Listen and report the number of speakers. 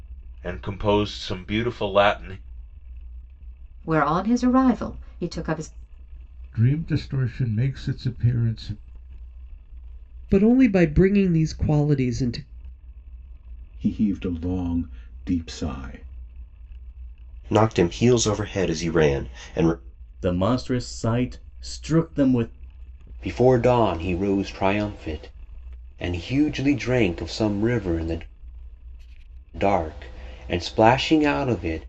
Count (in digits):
8